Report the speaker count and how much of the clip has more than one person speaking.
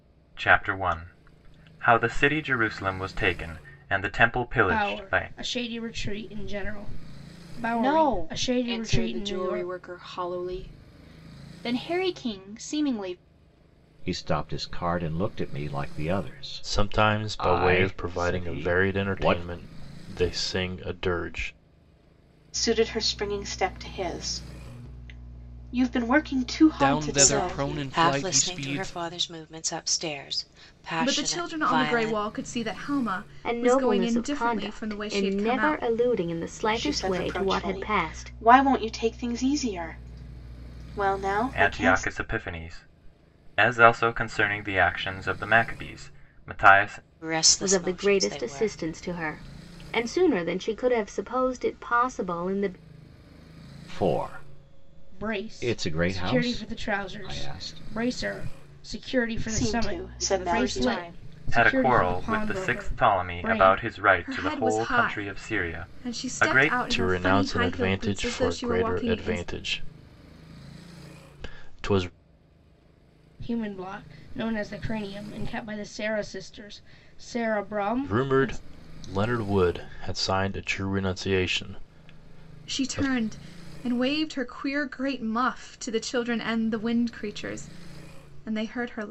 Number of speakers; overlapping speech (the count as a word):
ten, about 32%